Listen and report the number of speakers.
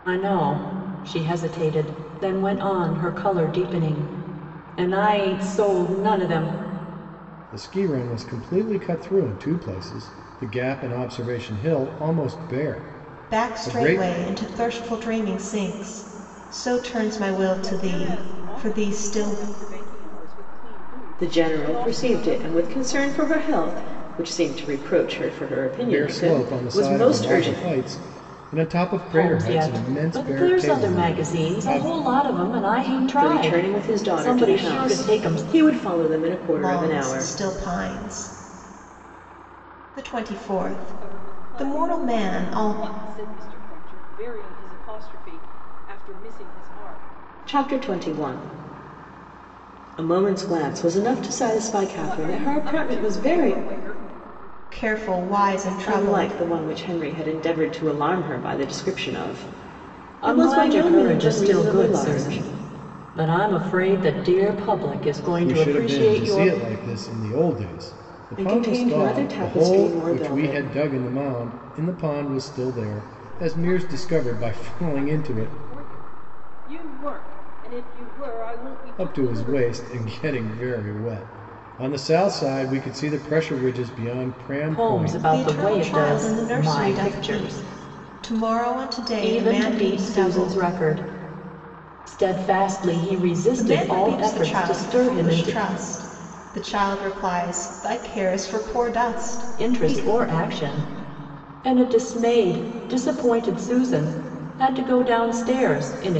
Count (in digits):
5